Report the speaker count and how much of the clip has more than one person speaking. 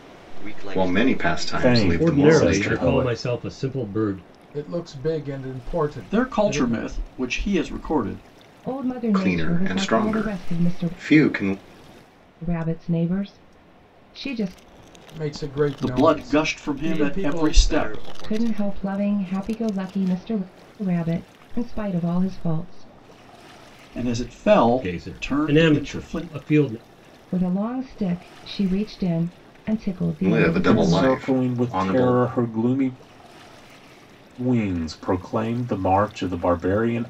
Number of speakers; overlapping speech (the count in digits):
7, about 32%